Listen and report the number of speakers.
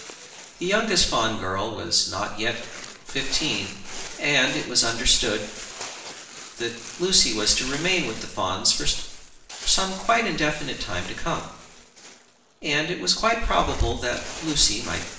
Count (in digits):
1